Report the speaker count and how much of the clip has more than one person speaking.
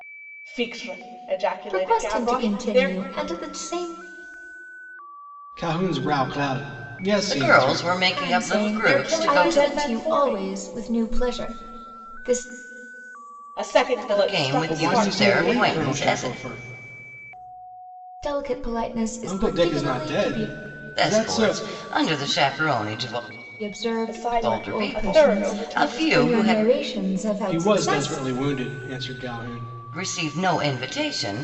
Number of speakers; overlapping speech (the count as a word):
four, about 38%